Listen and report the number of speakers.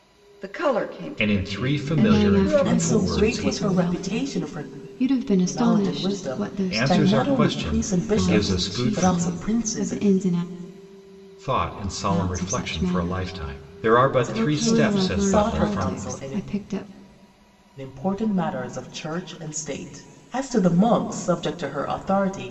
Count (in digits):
4